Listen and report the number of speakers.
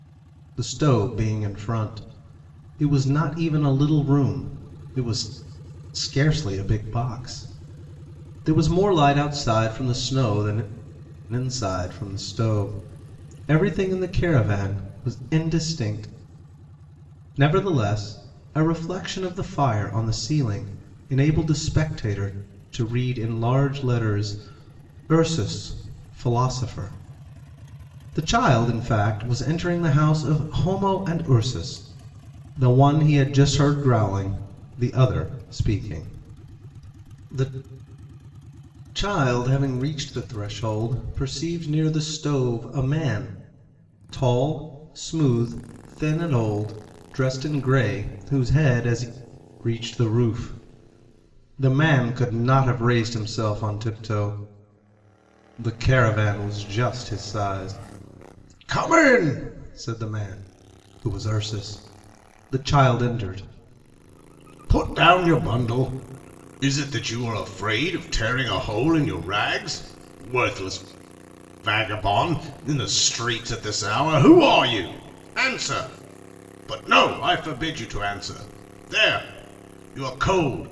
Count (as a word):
one